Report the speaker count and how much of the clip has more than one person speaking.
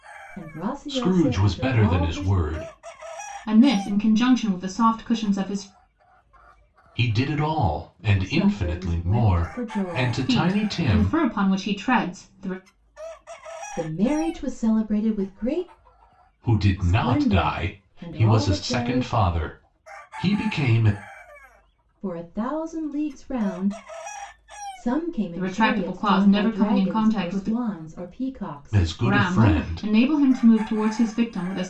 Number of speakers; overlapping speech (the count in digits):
3, about 32%